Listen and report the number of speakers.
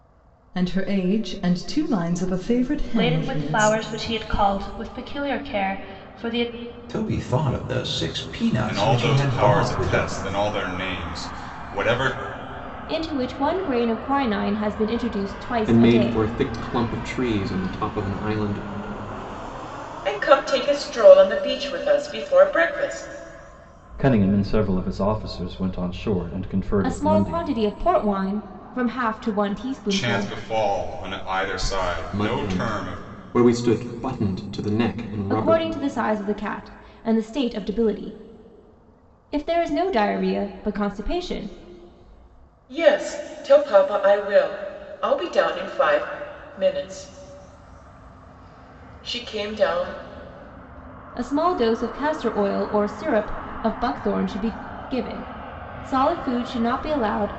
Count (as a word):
eight